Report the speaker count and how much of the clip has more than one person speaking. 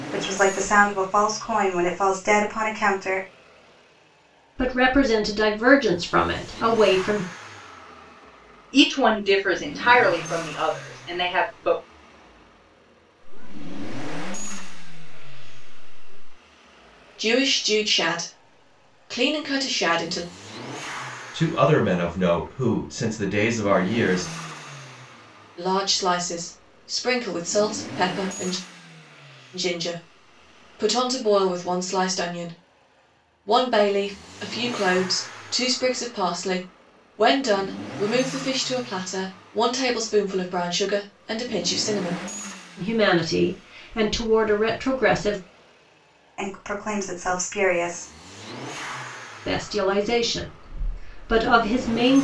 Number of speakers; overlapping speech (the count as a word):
six, no overlap